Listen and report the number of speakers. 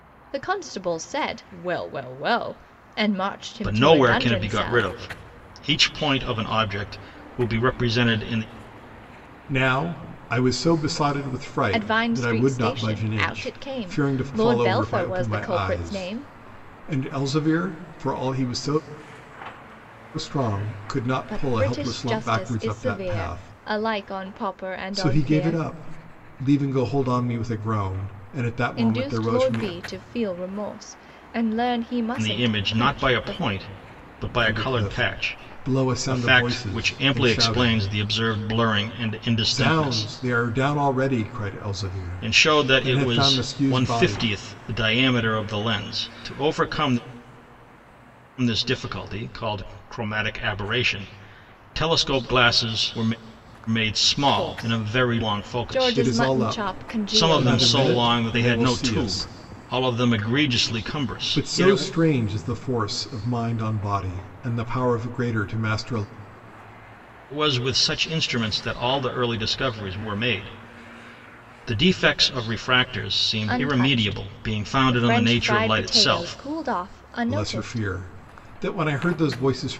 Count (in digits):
3